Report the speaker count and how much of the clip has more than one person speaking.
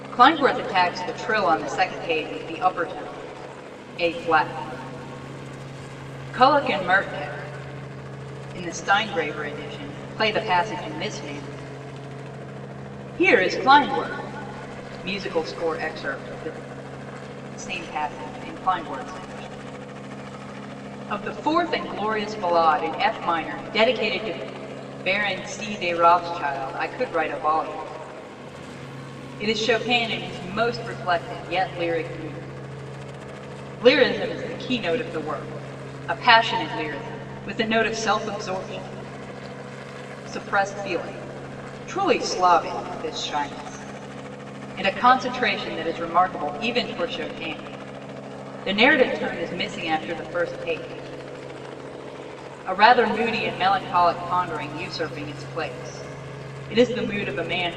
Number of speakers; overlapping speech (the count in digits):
1, no overlap